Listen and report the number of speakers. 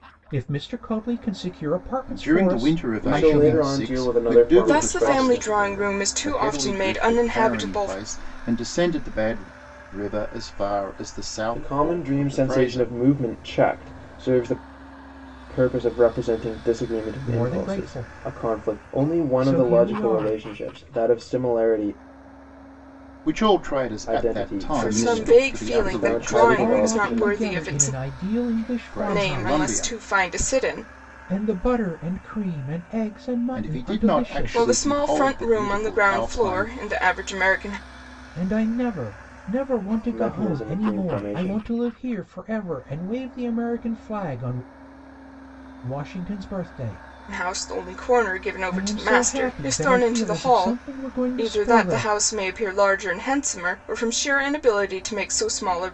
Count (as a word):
four